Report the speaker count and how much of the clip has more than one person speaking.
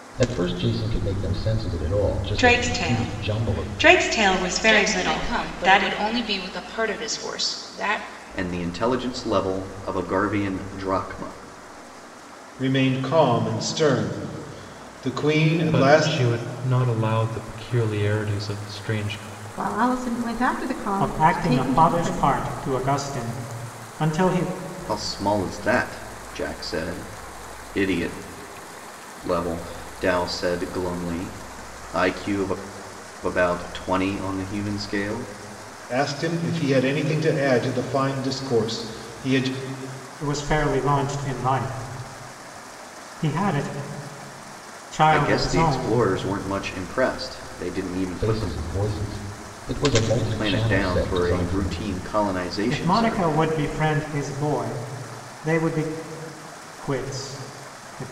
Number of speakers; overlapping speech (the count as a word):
eight, about 14%